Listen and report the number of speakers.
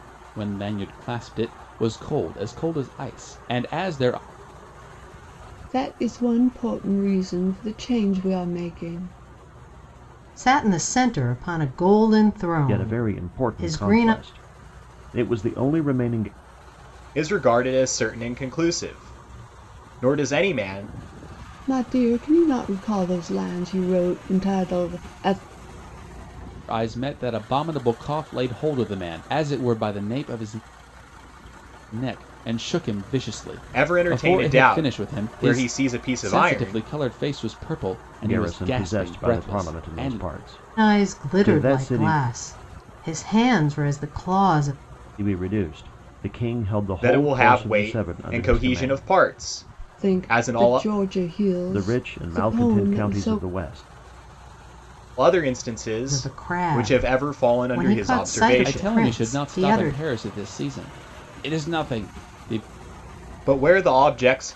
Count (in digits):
5